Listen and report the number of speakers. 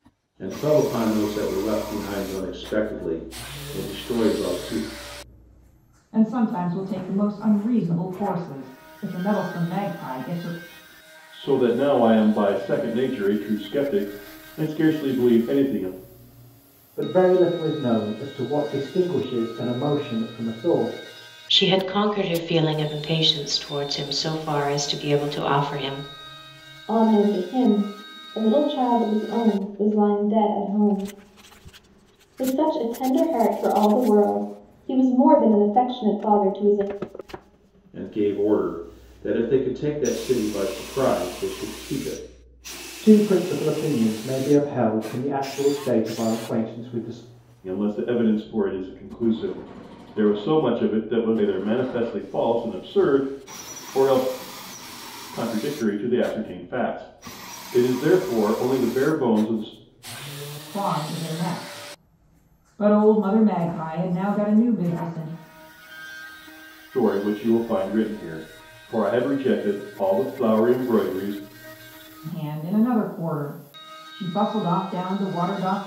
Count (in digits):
6